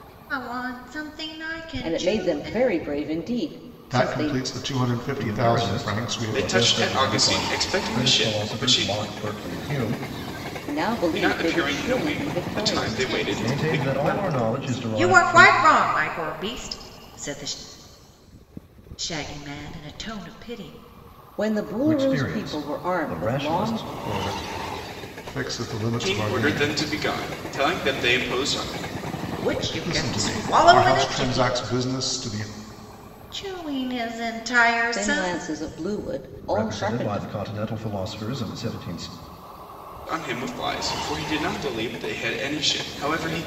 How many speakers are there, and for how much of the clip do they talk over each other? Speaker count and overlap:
five, about 36%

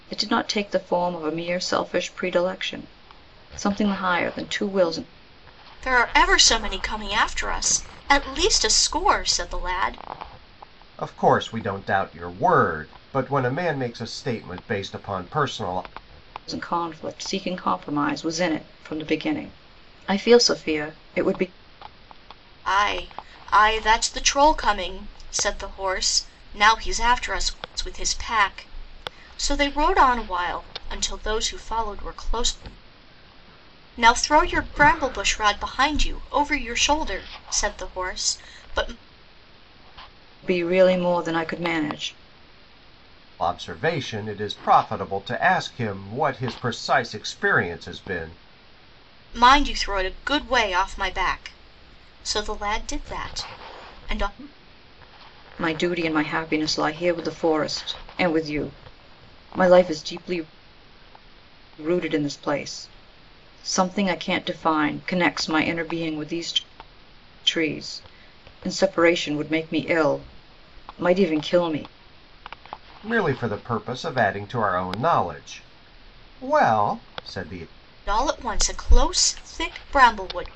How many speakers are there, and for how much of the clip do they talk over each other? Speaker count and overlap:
three, no overlap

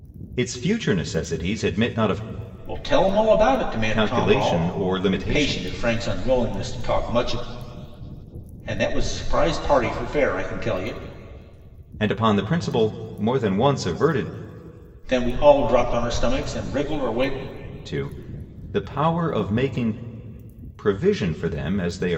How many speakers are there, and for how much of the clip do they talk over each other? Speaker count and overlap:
two, about 6%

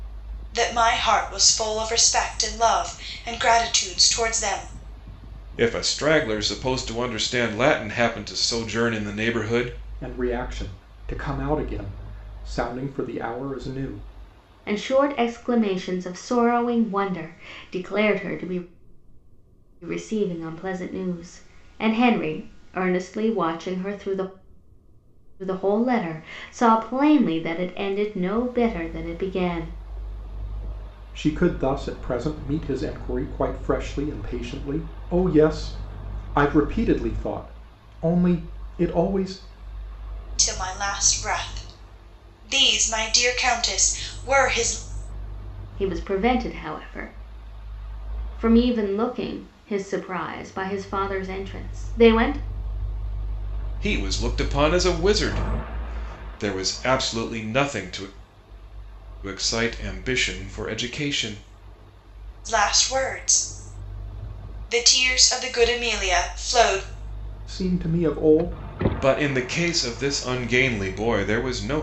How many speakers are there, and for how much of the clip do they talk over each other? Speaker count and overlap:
four, no overlap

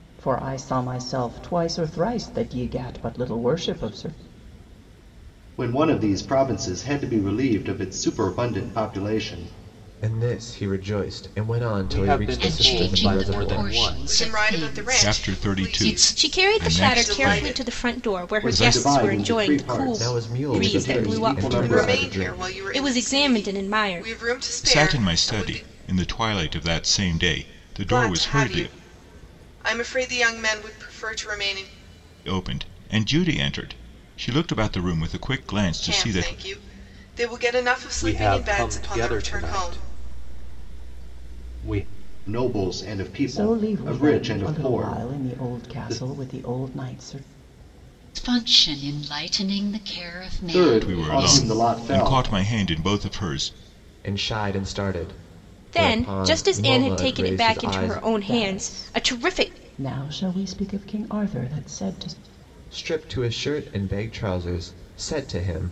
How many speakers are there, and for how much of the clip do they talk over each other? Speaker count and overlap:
eight, about 38%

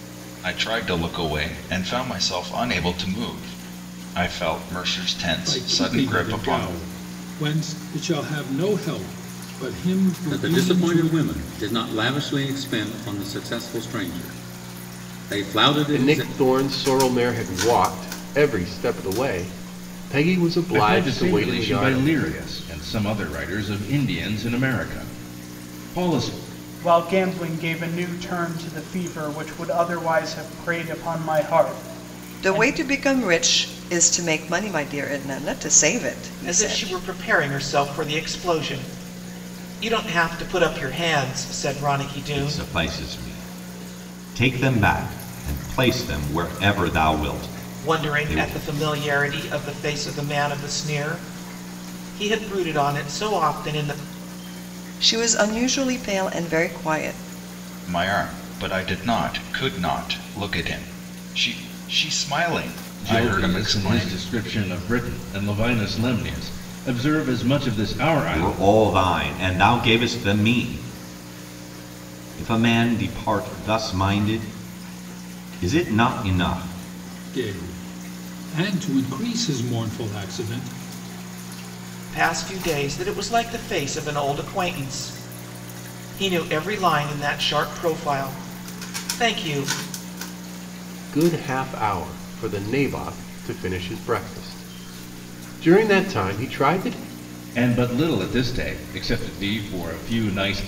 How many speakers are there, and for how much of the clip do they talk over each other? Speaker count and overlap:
nine, about 8%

